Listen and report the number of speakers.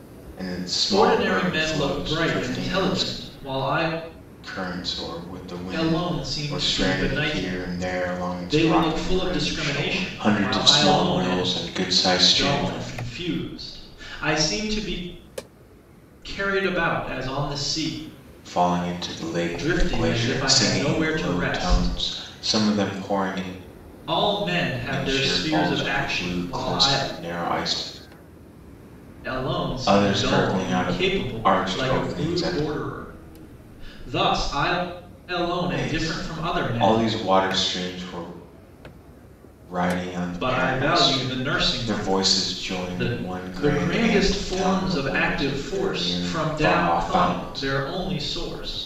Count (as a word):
two